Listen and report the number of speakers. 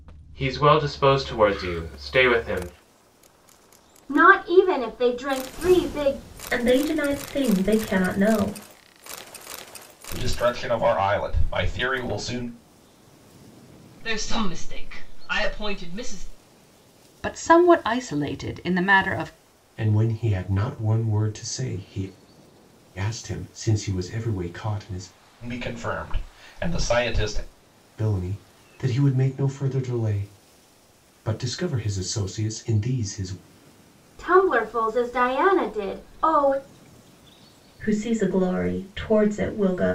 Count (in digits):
7